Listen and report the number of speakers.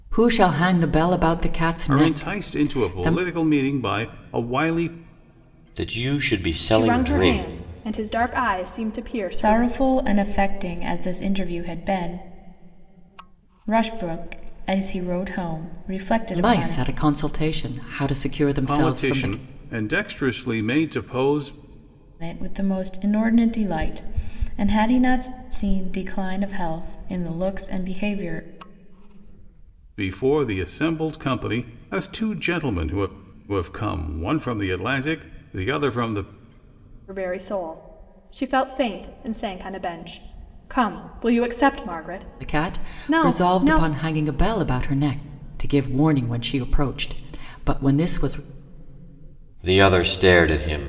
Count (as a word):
five